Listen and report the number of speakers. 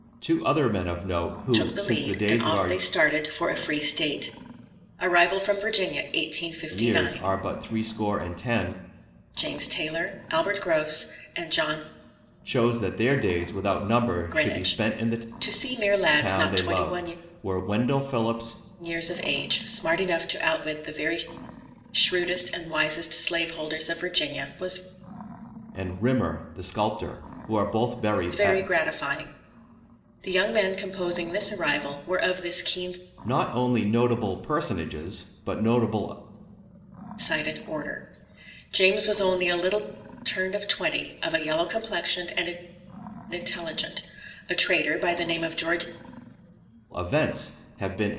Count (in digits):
2